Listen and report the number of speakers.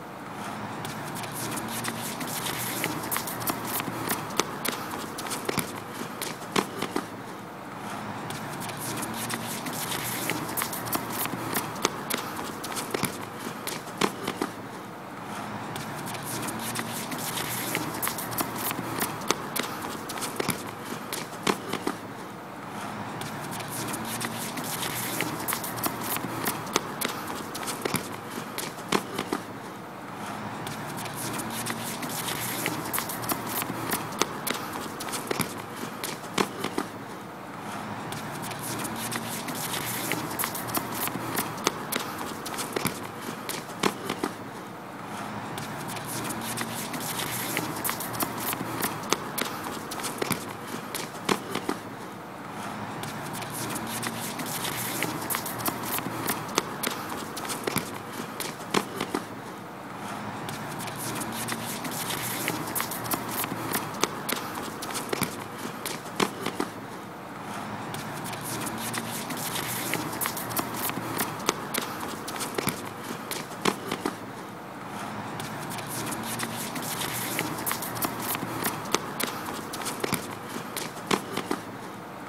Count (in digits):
0